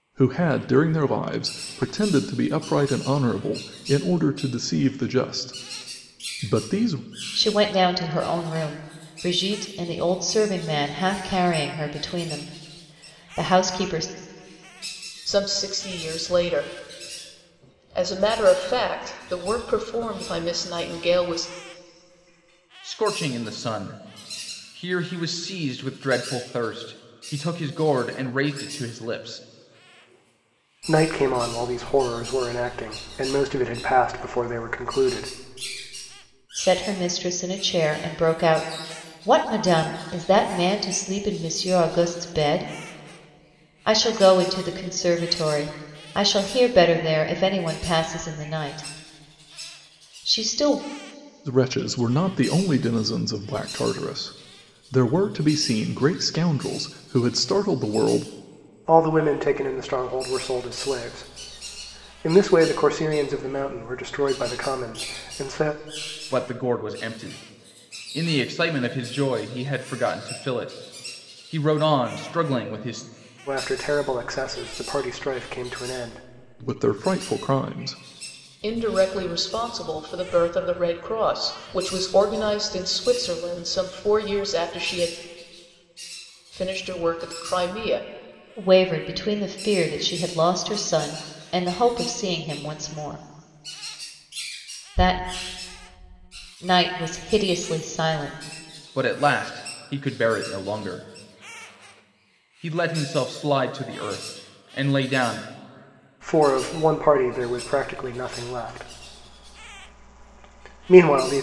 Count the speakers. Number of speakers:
five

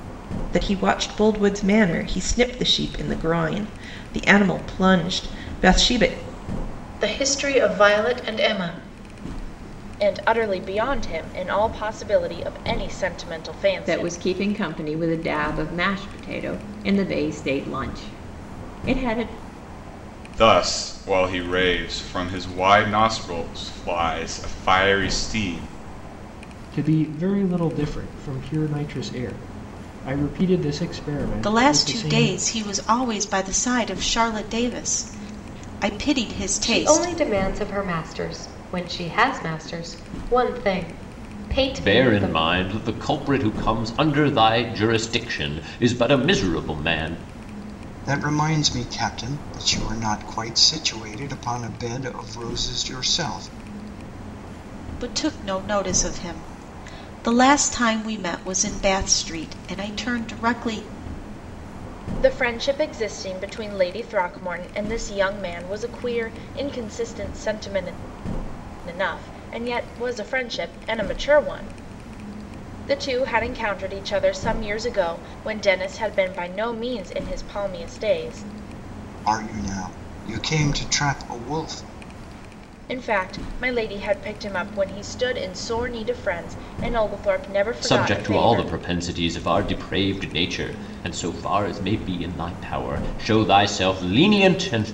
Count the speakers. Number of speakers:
ten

